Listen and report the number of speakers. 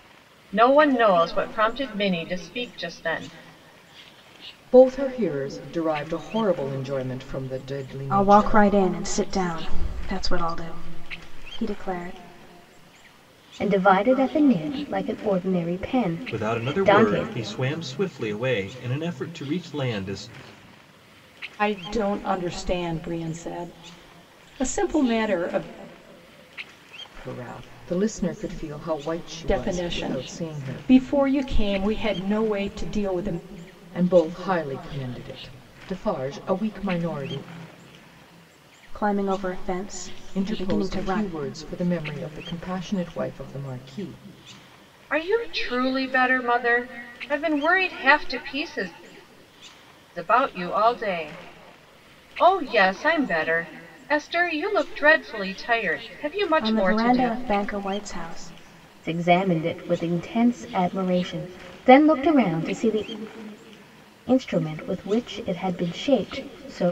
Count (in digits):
6